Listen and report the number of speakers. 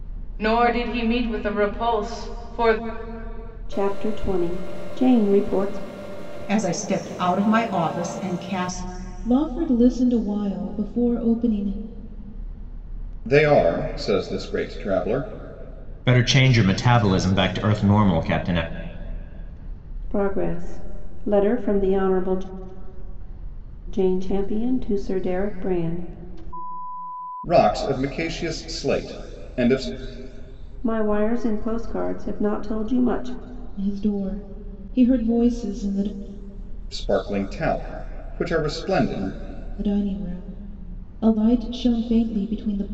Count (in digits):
6